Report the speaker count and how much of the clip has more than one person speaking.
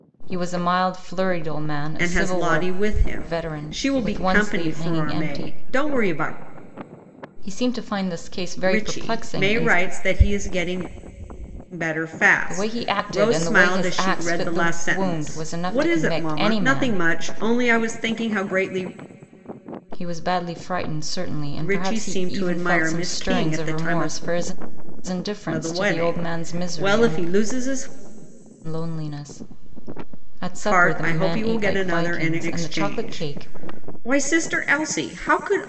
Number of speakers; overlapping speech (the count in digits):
2, about 44%